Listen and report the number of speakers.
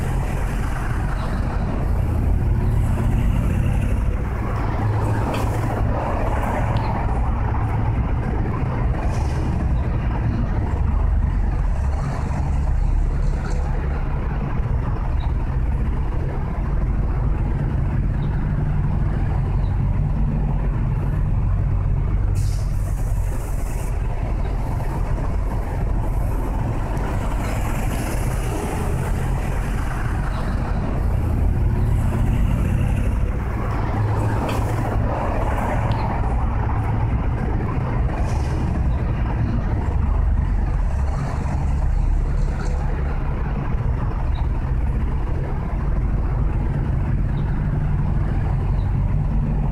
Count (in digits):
0